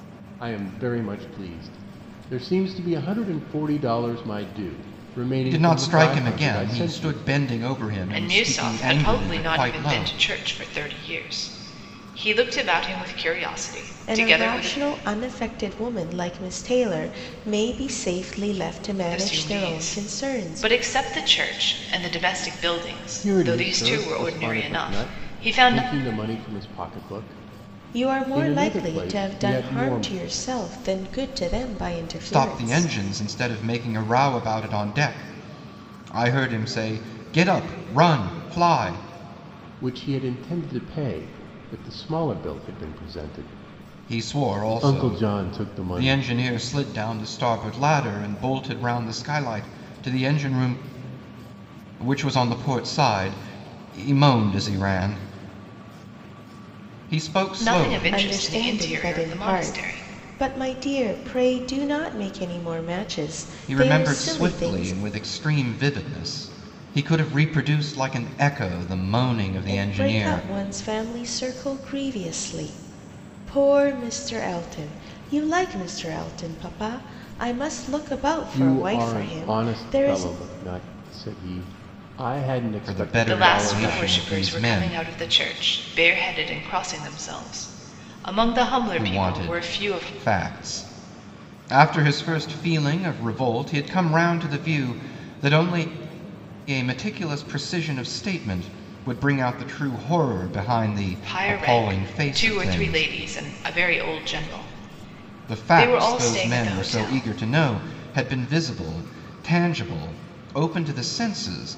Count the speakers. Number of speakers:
4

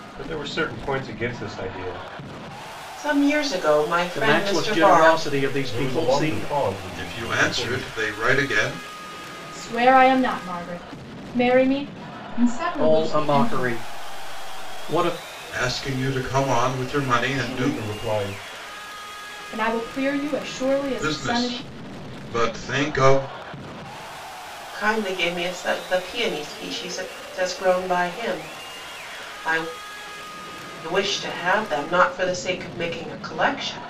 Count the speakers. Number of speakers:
7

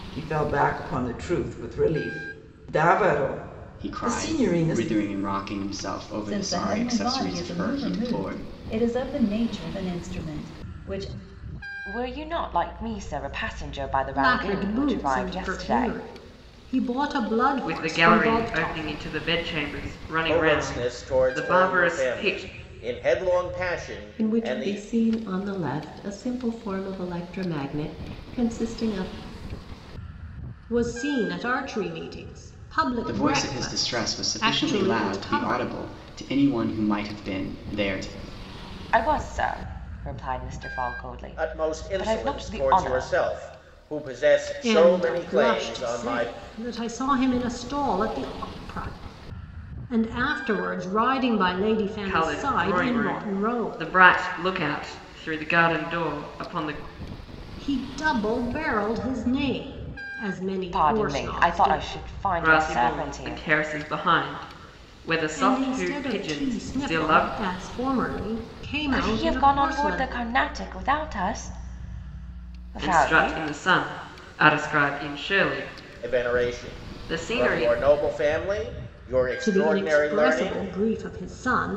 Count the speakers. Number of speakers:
8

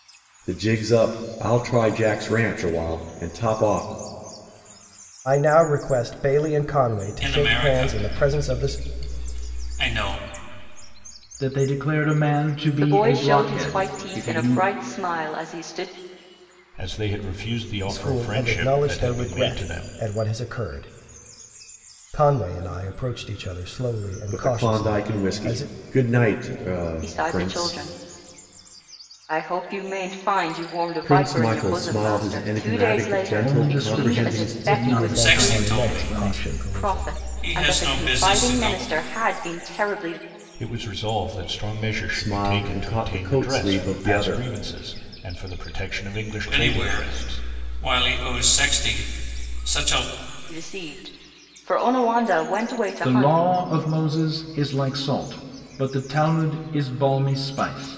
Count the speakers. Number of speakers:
6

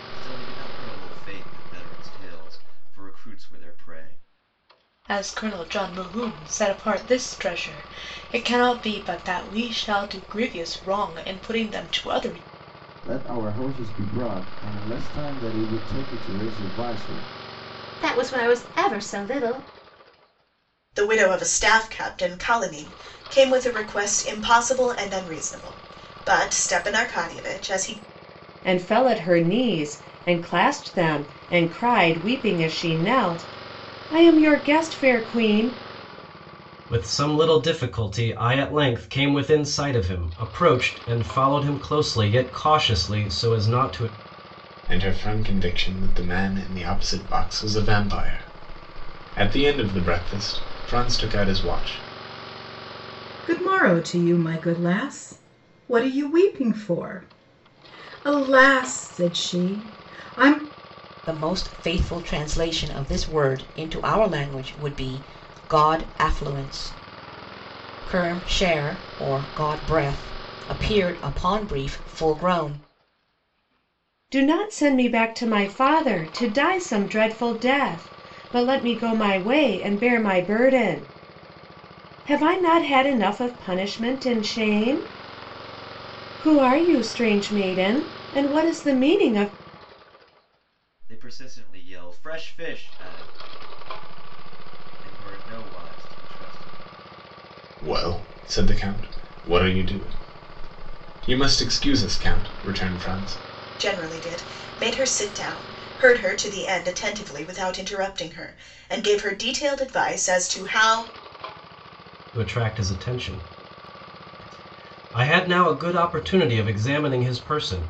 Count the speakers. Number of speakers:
10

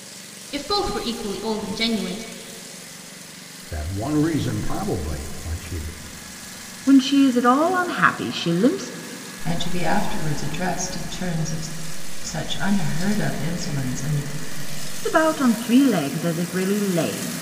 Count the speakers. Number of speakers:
4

